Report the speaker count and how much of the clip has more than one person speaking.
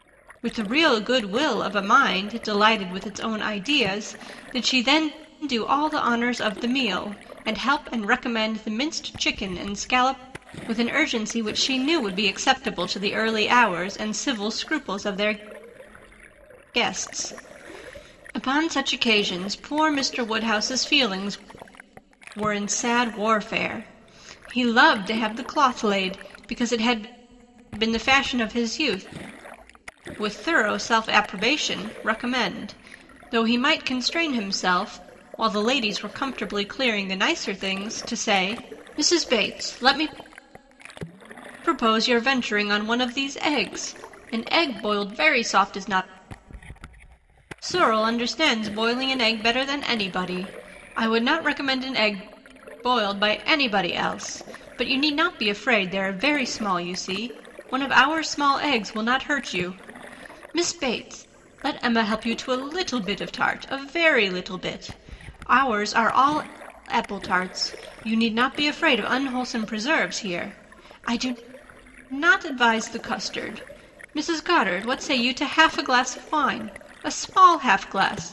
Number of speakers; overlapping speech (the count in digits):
1, no overlap